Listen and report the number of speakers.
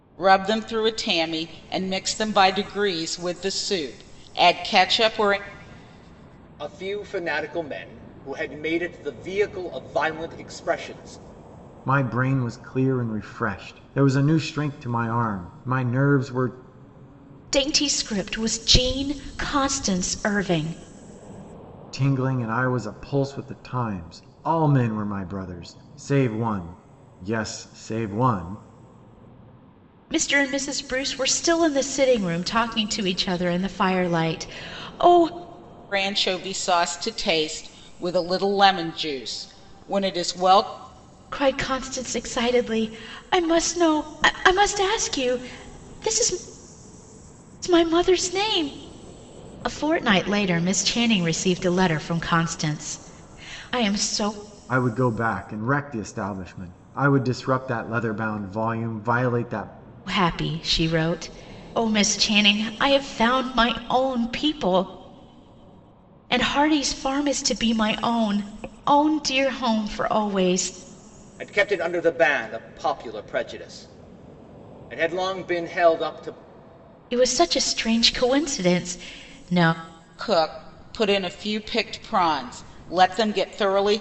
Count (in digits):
4